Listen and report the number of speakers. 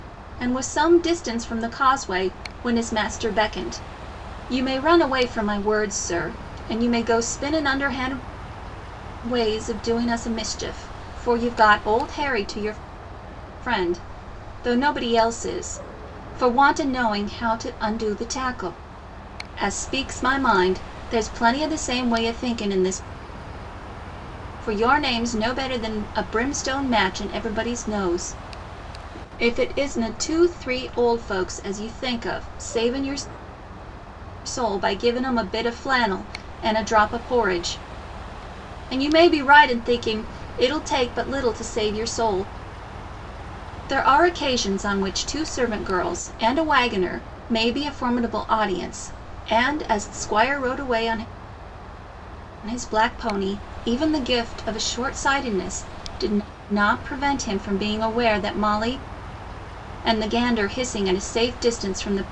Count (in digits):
1